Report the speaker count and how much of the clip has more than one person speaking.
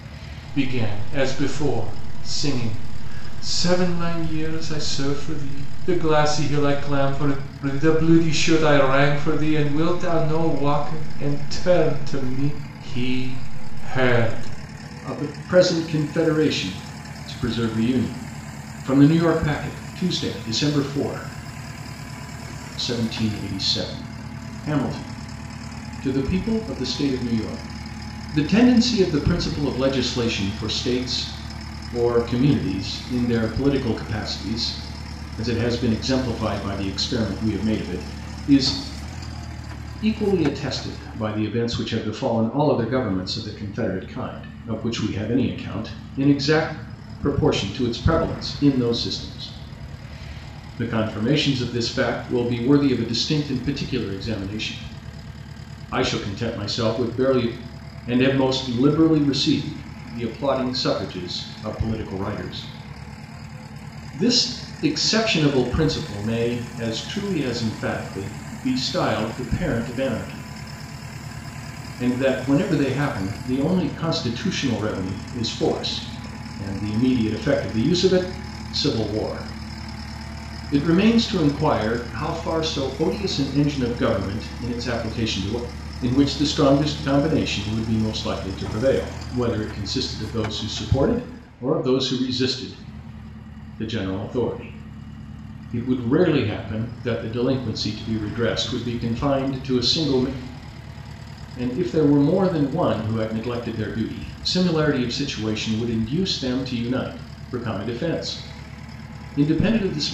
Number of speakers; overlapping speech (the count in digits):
1, no overlap